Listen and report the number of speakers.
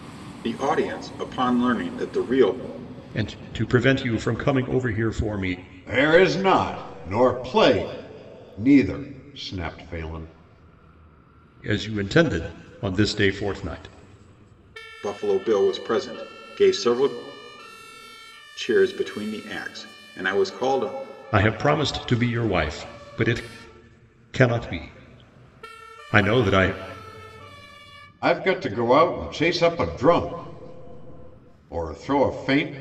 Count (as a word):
three